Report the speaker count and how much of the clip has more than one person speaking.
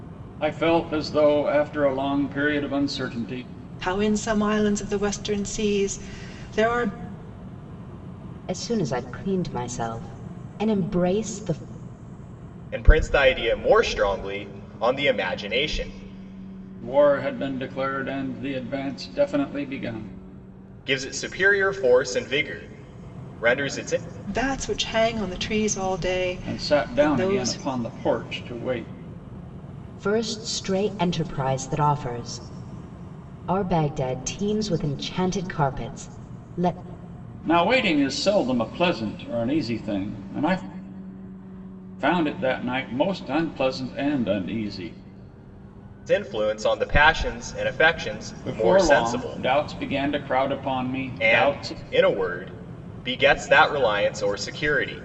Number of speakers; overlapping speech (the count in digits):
4, about 5%